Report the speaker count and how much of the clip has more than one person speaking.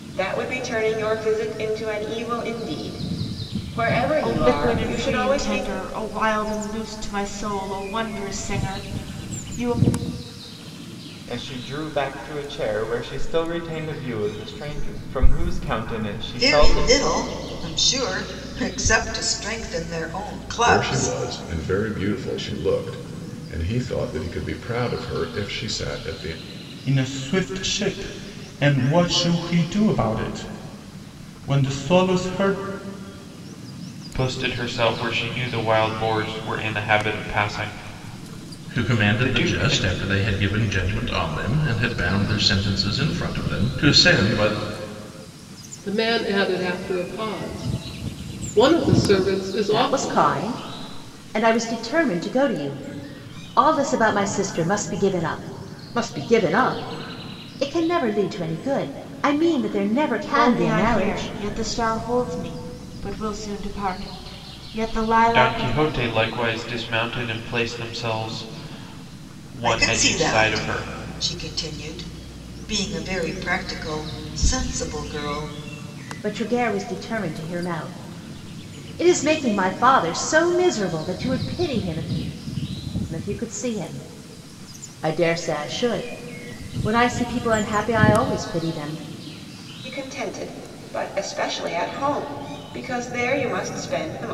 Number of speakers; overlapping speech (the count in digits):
10, about 8%